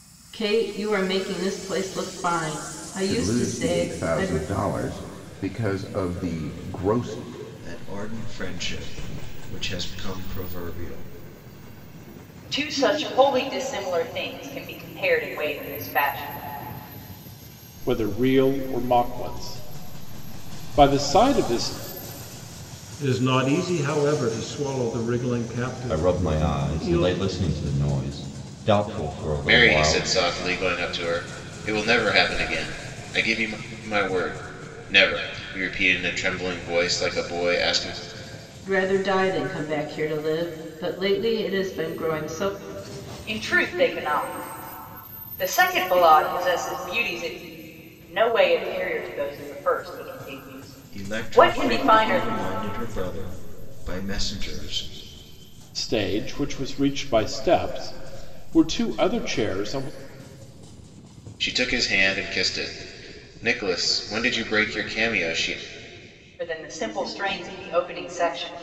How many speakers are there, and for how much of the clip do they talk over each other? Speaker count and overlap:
eight, about 7%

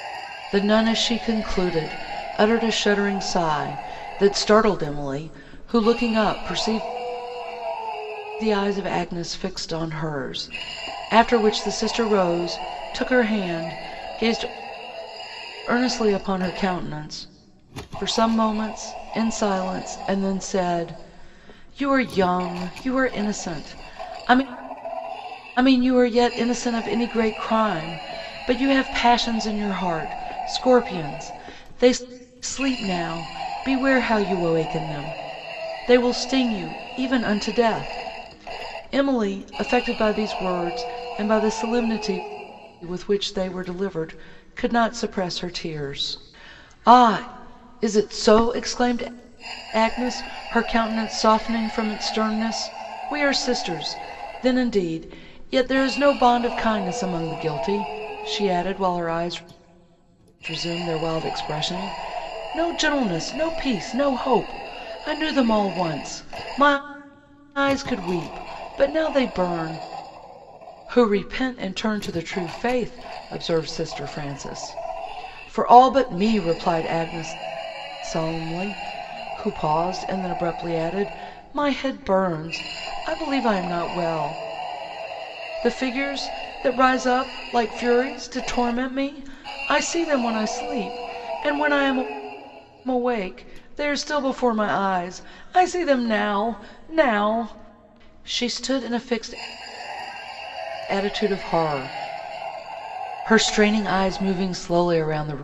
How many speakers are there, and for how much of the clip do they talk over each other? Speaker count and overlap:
one, no overlap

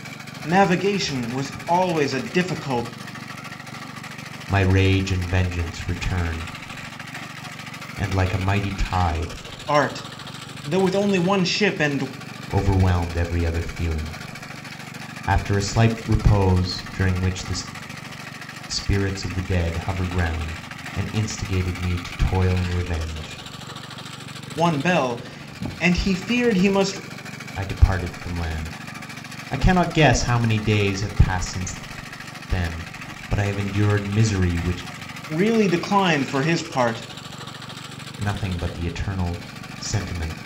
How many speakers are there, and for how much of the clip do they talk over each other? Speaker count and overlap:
two, no overlap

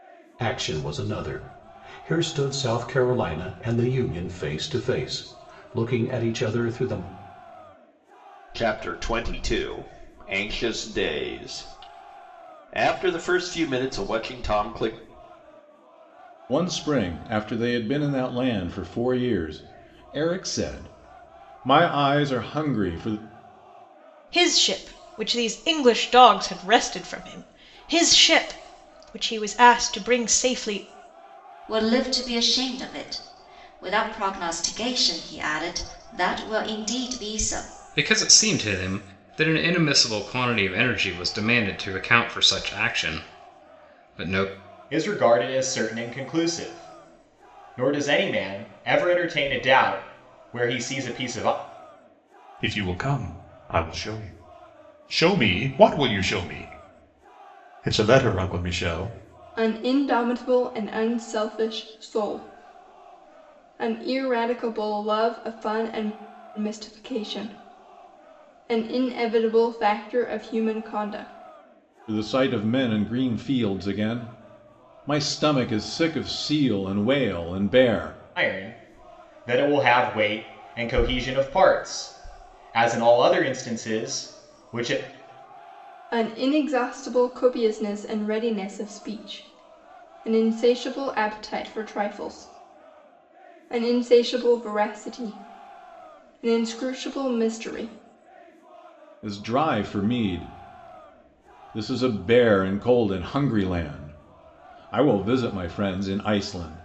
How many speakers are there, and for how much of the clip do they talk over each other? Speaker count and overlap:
nine, no overlap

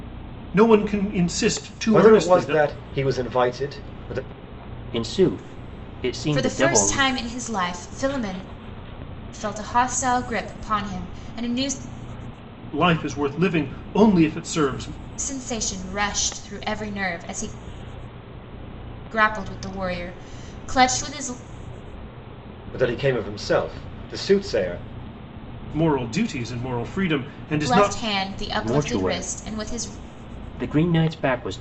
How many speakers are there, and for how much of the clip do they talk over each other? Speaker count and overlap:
four, about 10%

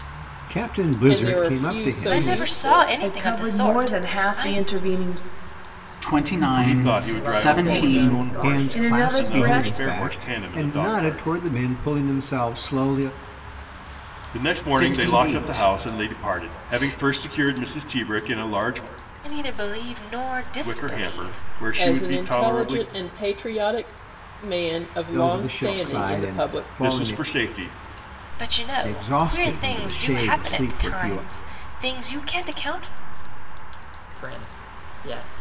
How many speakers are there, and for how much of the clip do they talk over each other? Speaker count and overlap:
seven, about 49%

